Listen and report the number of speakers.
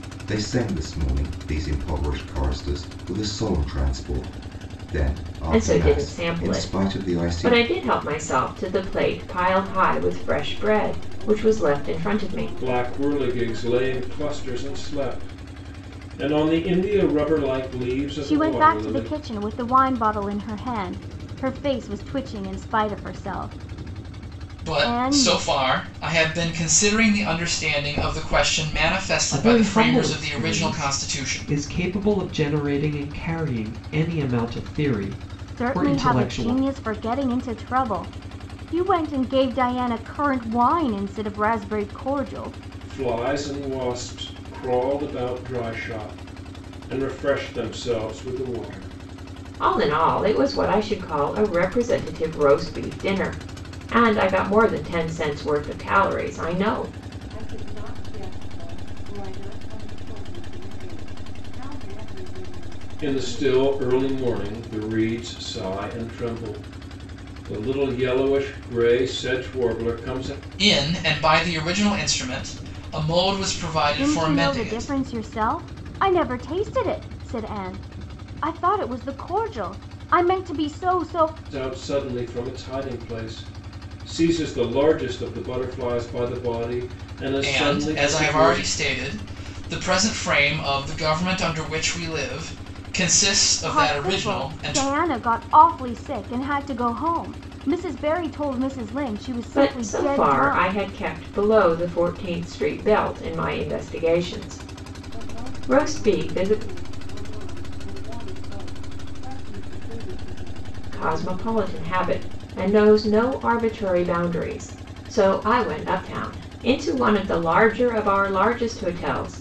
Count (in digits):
7